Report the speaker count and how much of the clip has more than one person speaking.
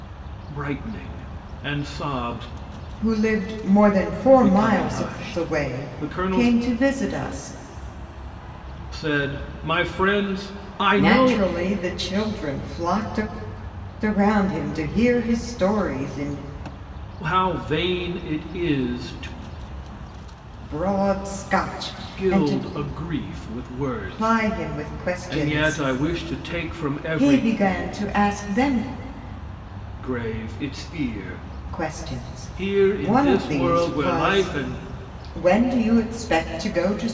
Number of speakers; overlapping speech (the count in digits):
2, about 17%